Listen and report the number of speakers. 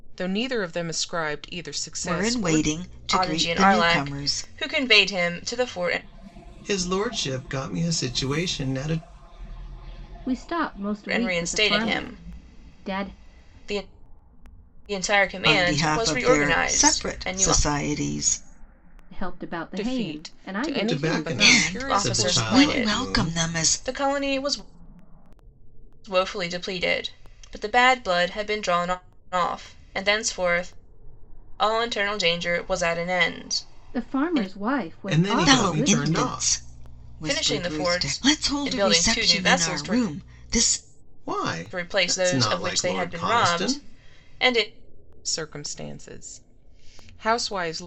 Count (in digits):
5